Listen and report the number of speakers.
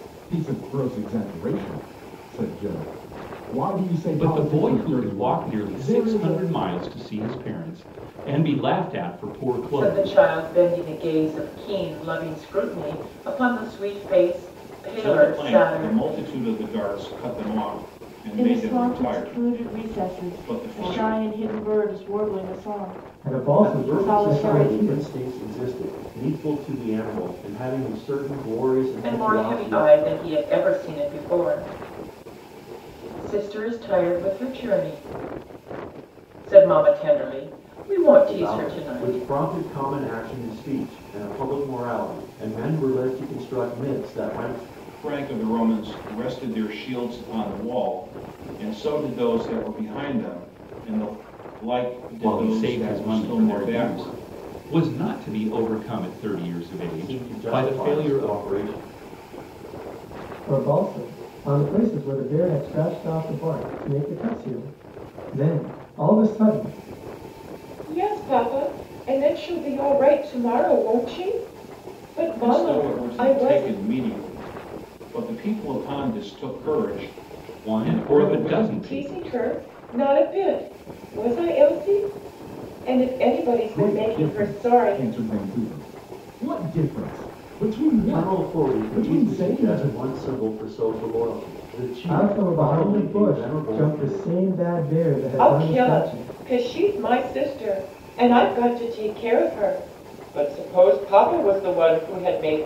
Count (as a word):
seven